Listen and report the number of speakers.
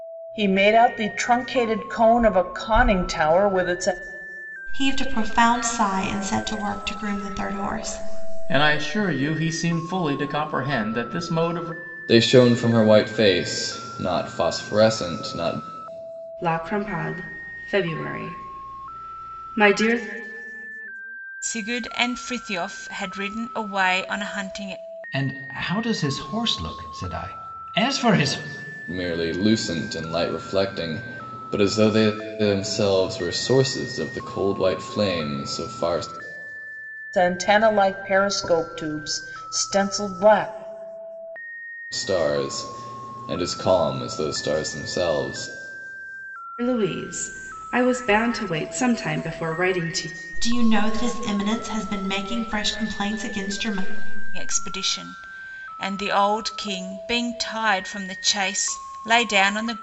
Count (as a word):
seven